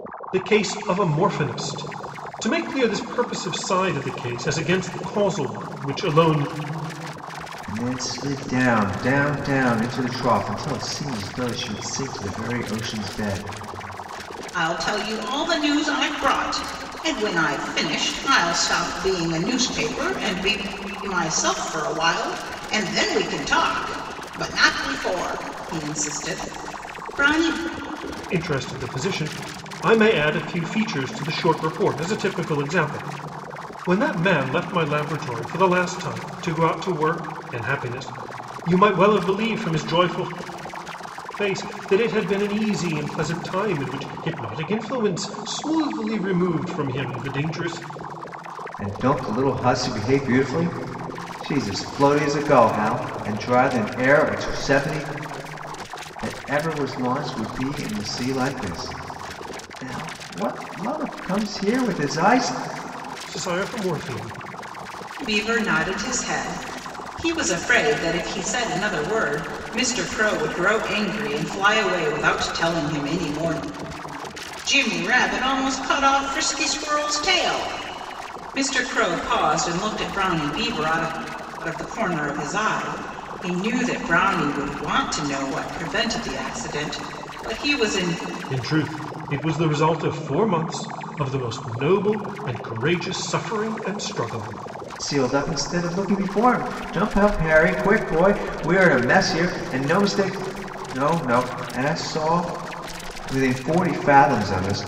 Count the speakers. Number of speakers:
three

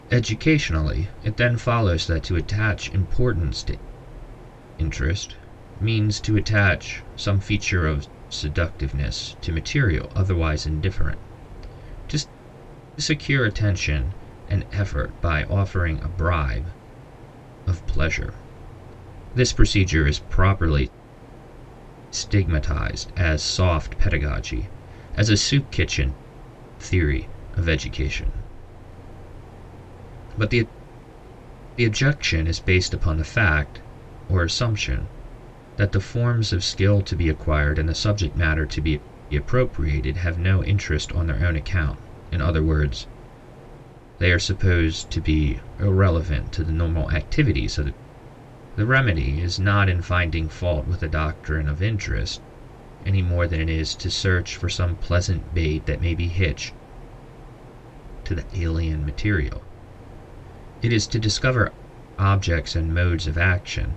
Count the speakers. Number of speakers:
one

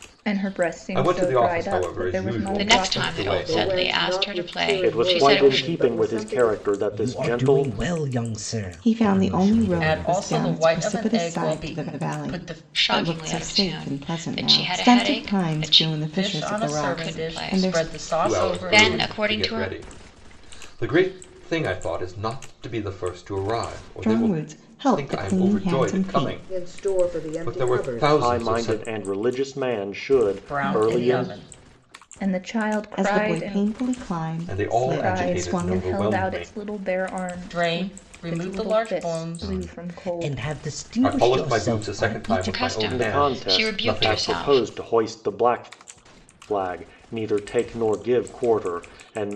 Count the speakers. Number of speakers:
eight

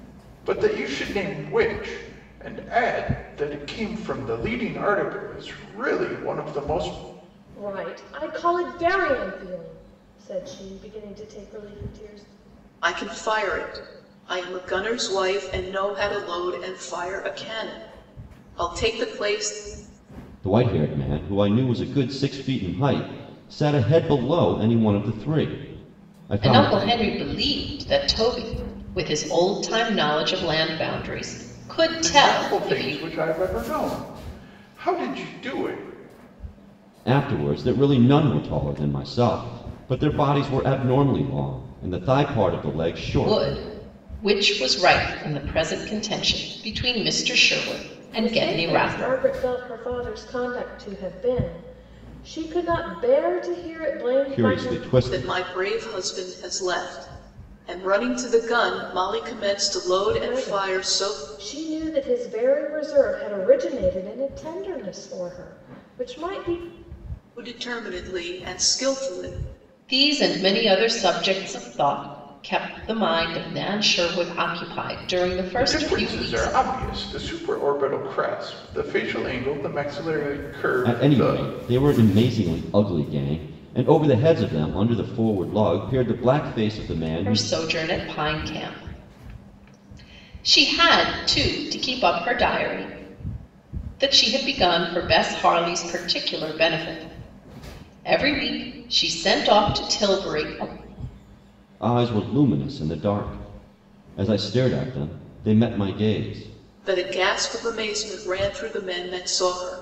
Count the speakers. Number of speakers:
five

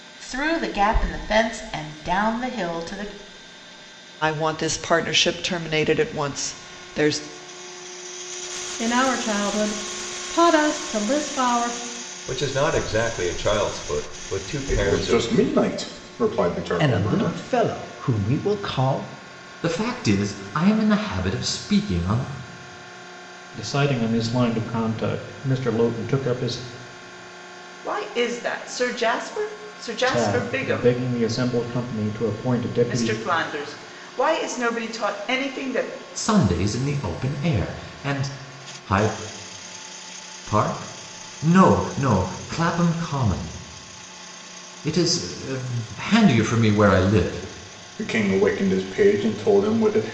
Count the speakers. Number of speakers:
nine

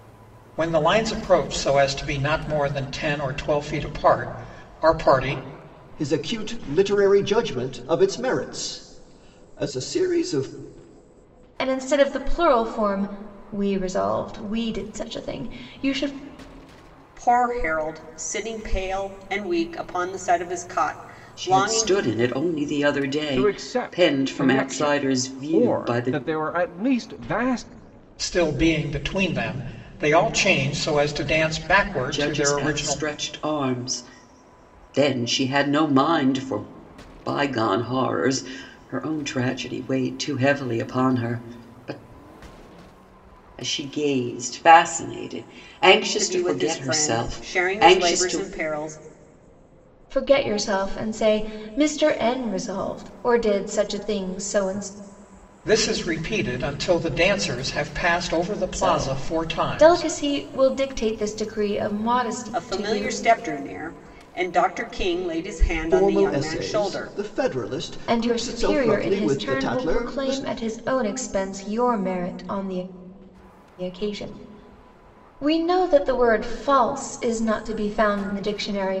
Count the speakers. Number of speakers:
six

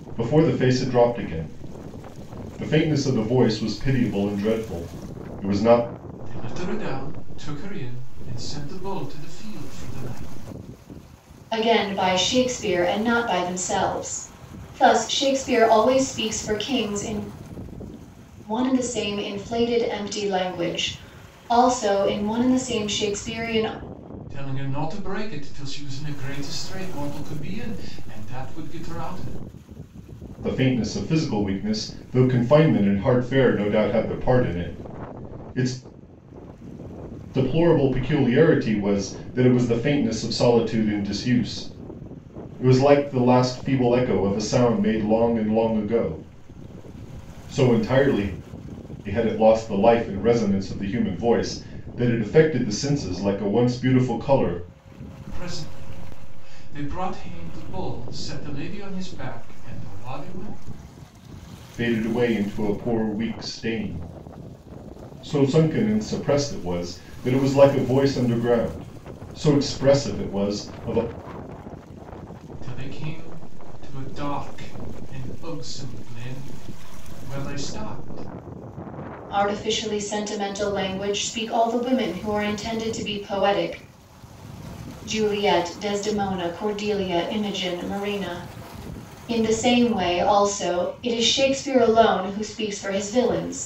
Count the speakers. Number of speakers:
three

